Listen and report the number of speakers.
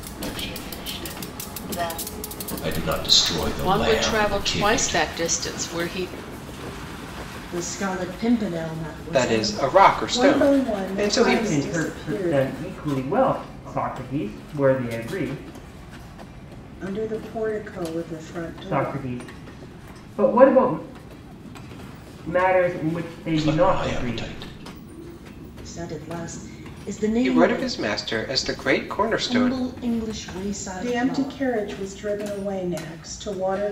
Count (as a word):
seven